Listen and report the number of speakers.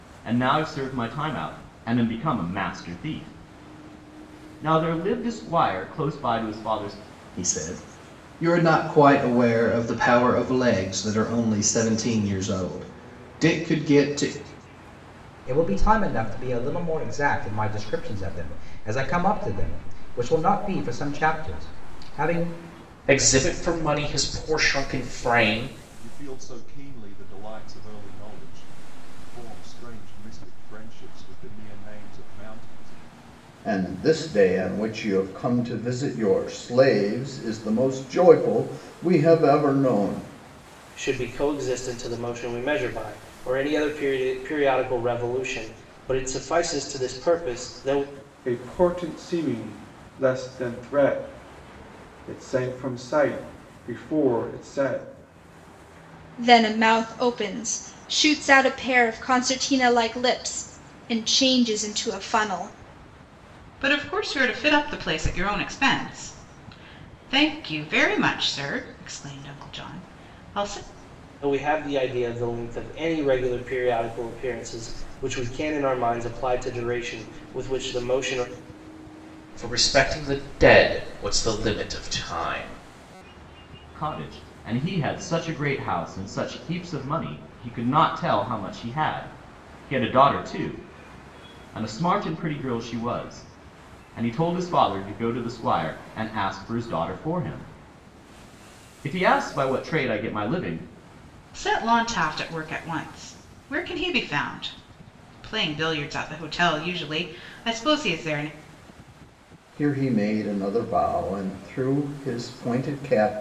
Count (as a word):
ten